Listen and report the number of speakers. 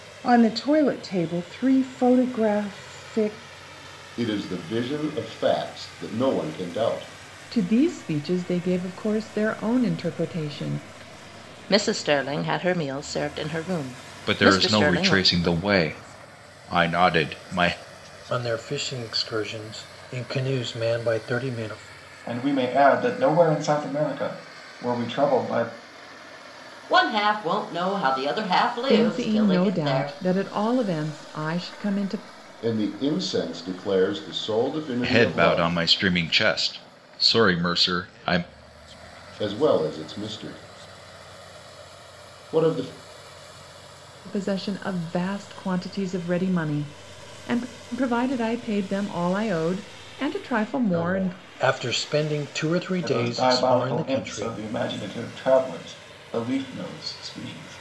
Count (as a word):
eight